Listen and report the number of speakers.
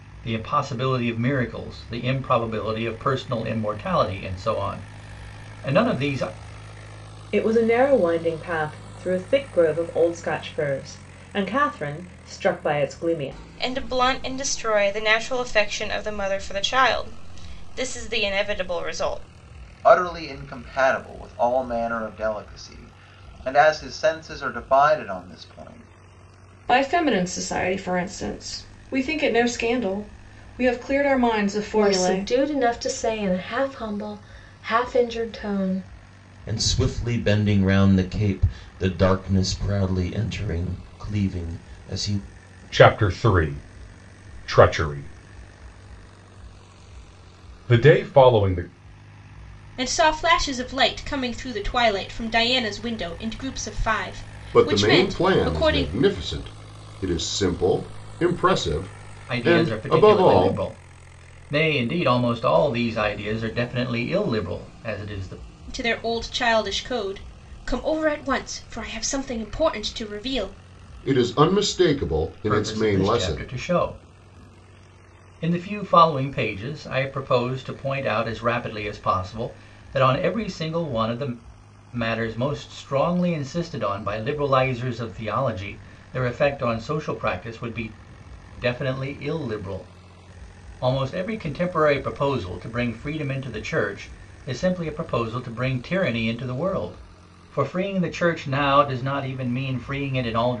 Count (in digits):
10